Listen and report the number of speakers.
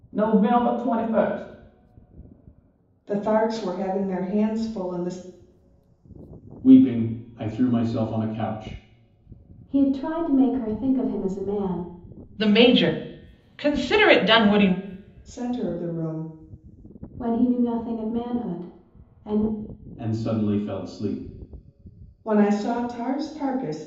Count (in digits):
5